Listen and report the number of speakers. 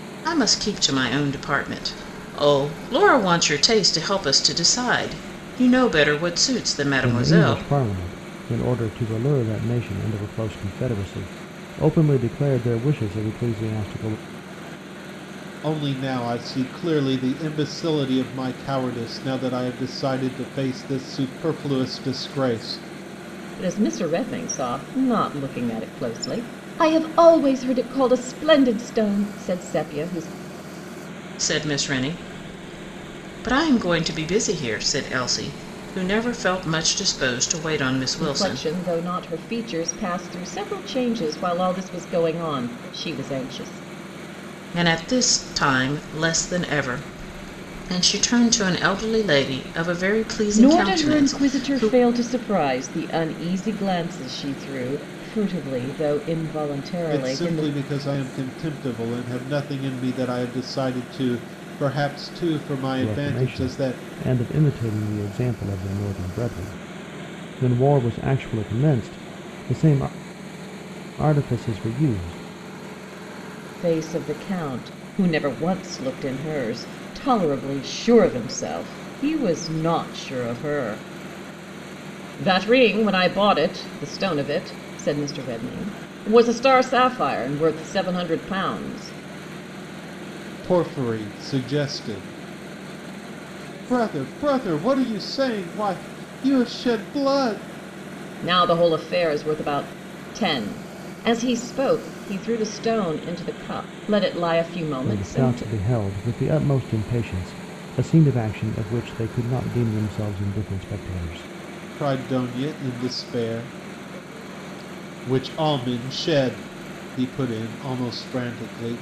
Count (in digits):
4